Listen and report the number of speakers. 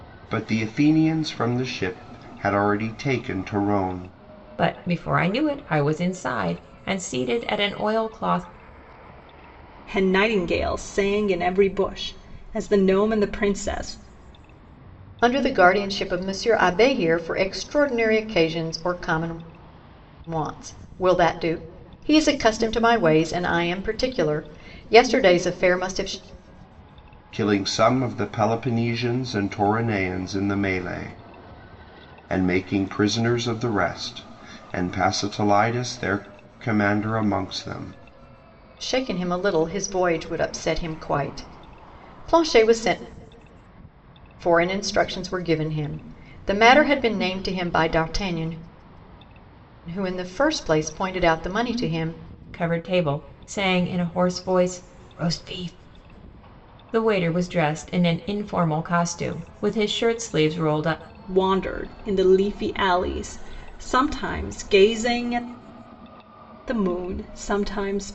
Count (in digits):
4